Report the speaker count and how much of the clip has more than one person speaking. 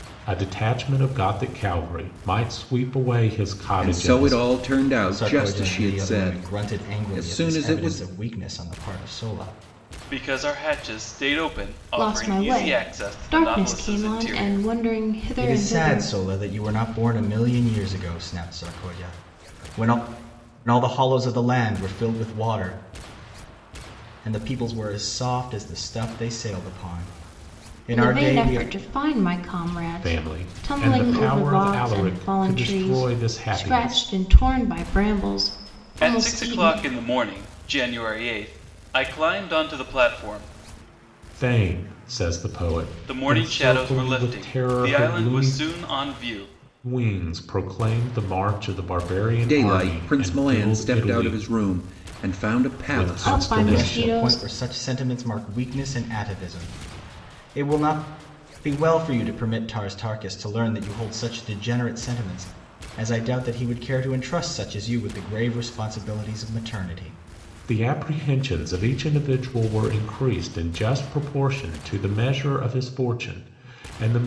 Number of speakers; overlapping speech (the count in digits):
5, about 26%